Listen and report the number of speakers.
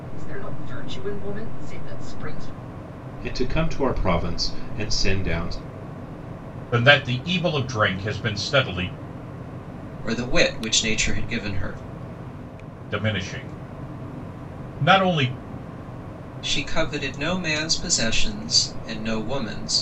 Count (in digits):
4